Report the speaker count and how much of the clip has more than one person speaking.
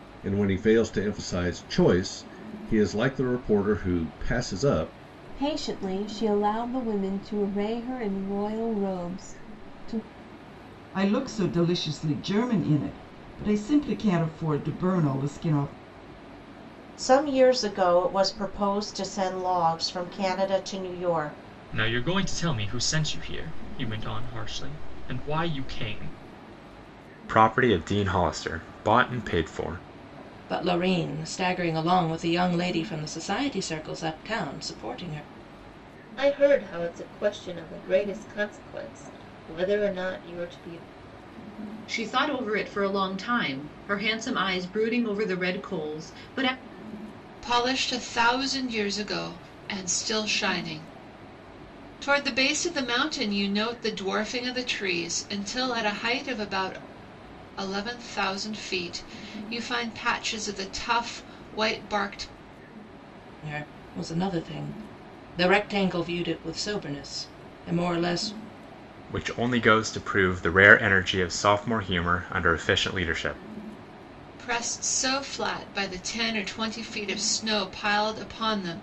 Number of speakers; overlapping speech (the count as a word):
ten, no overlap